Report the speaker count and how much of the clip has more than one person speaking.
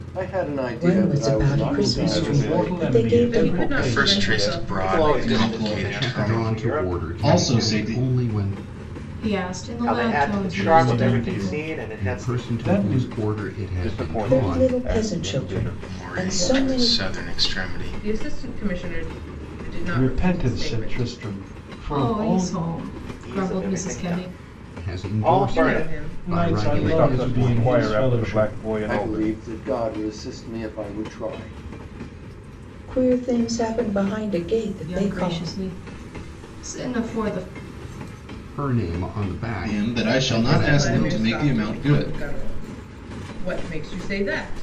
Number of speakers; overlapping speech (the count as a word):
ten, about 56%